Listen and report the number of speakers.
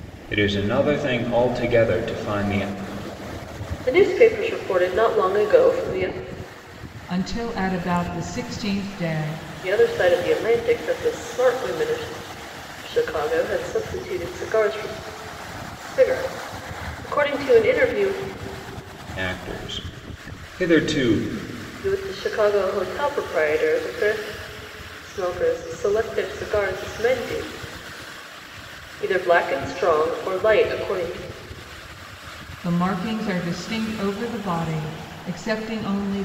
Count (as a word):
three